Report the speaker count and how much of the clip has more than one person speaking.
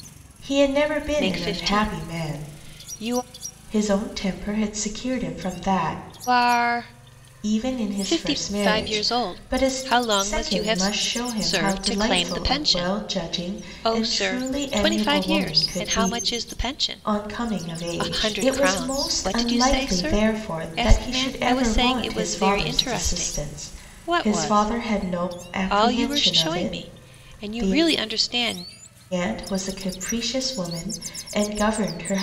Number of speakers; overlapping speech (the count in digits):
2, about 56%